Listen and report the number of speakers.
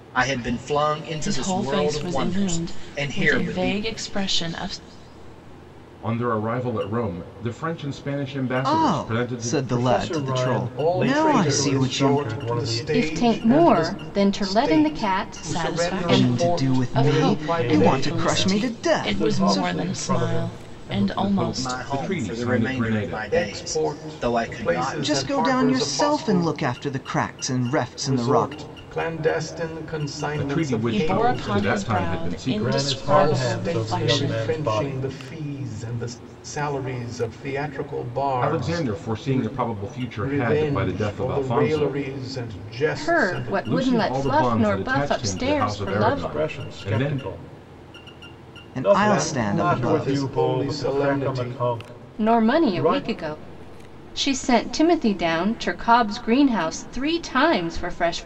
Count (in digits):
7